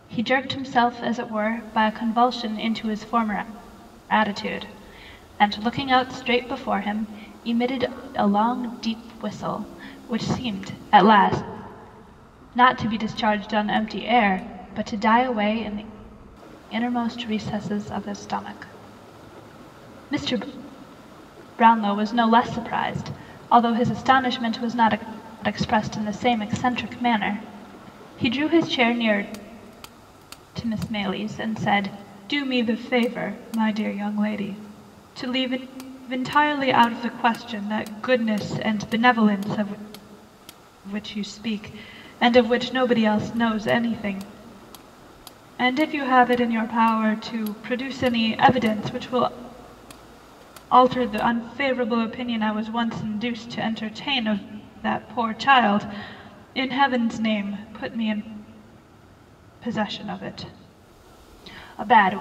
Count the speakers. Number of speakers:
1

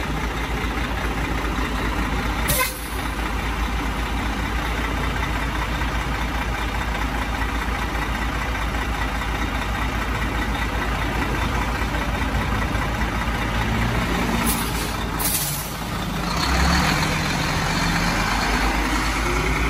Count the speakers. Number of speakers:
0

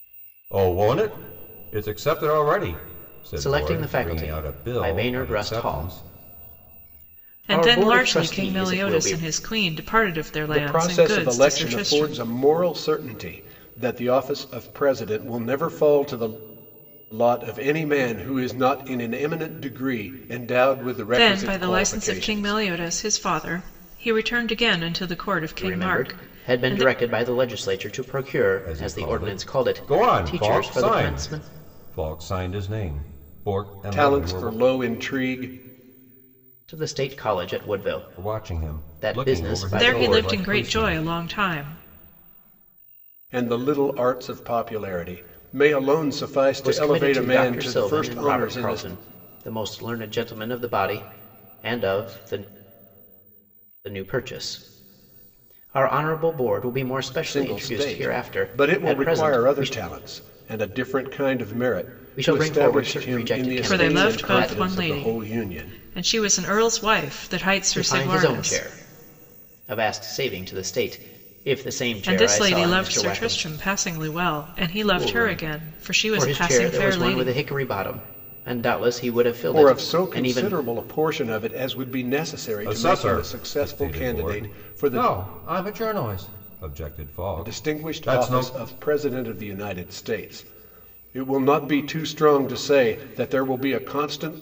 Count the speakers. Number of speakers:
4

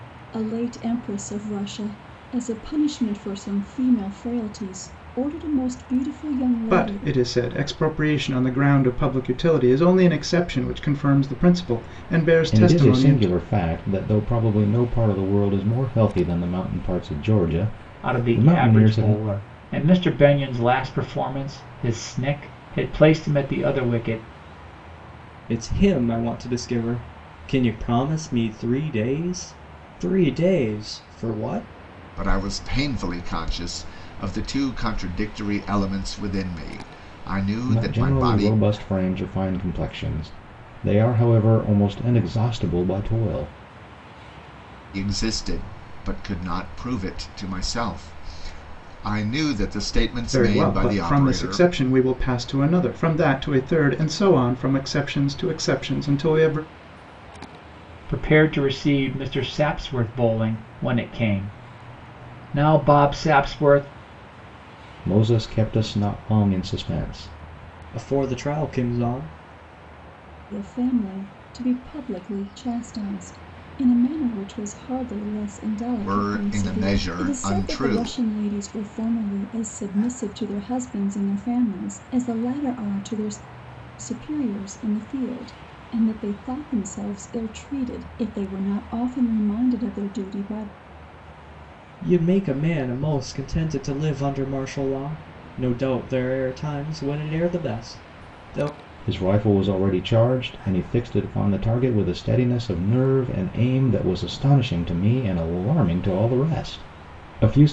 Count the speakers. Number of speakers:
6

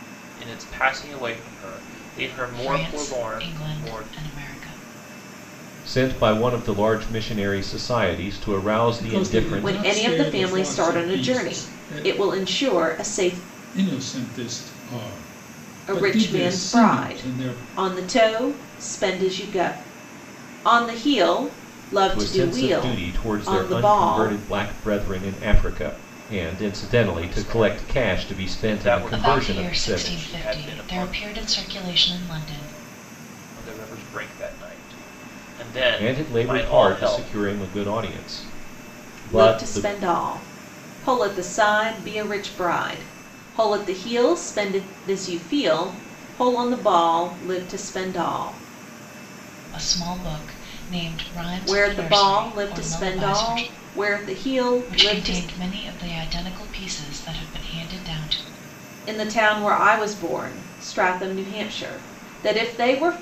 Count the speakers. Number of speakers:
5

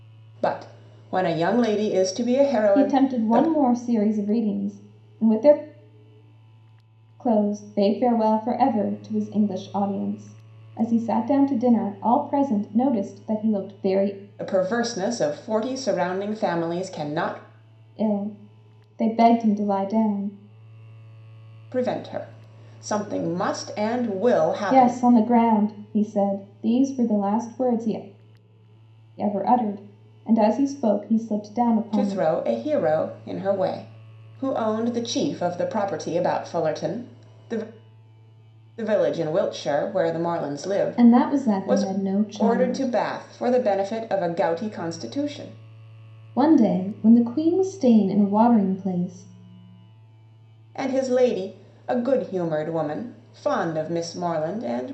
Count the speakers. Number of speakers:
2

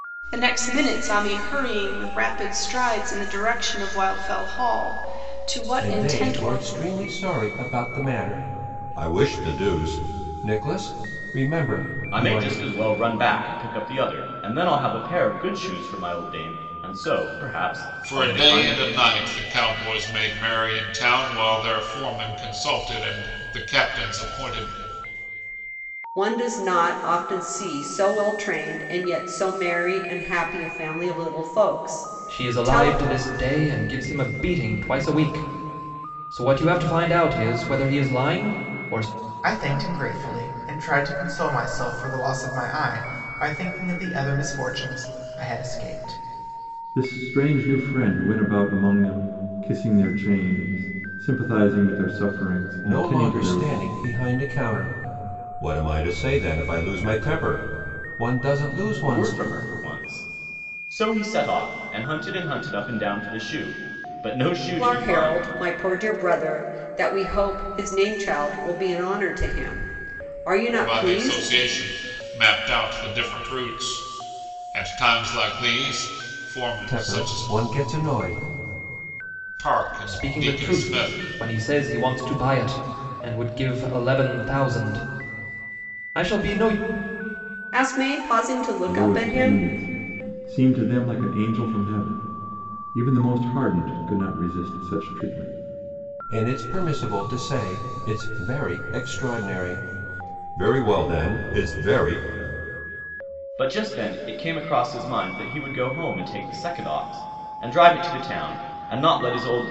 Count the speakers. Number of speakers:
8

